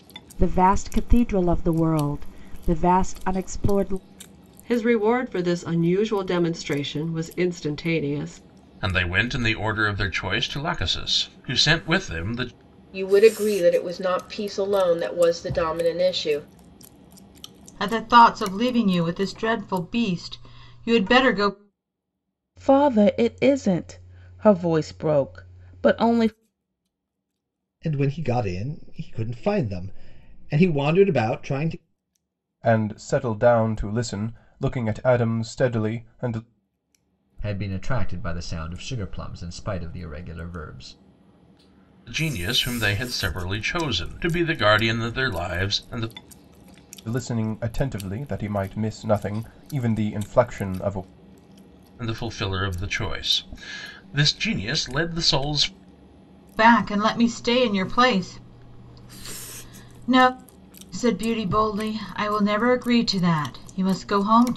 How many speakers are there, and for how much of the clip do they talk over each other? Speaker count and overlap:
9, no overlap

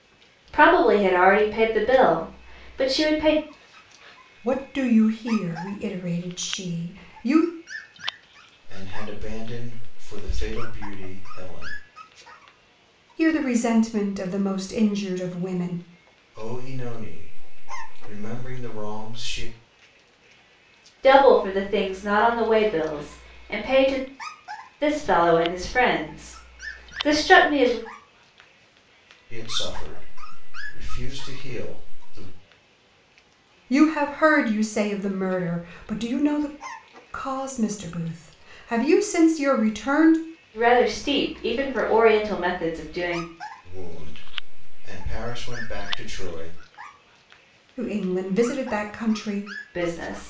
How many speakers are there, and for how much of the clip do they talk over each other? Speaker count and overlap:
3, no overlap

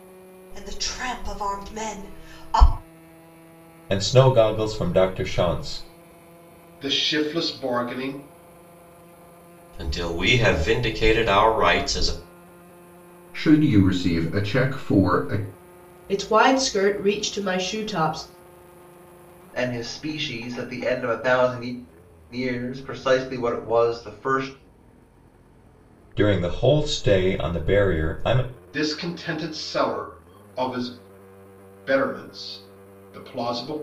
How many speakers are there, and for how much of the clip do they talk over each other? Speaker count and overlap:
7, no overlap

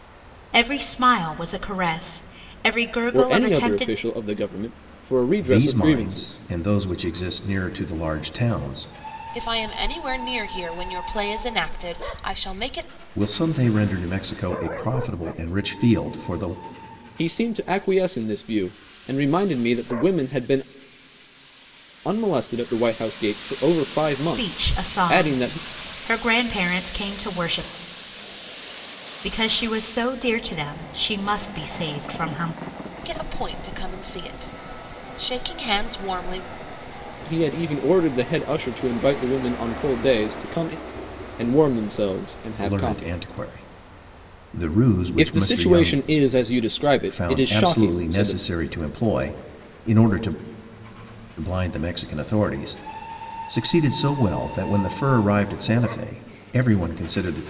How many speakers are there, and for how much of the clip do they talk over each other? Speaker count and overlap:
4, about 11%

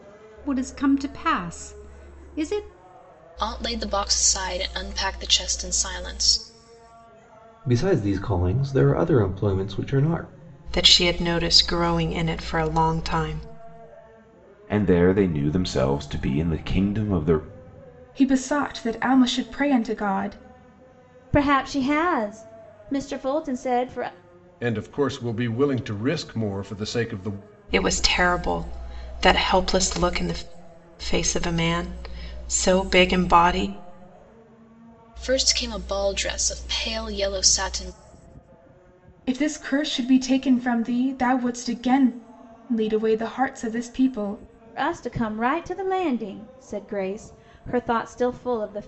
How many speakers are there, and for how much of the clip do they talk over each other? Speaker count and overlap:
8, no overlap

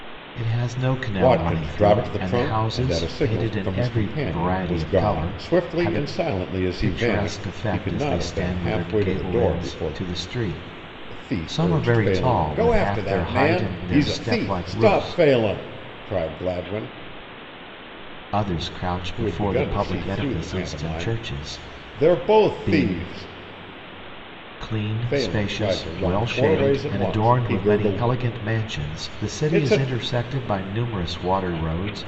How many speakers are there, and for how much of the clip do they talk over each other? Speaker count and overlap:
2, about 62%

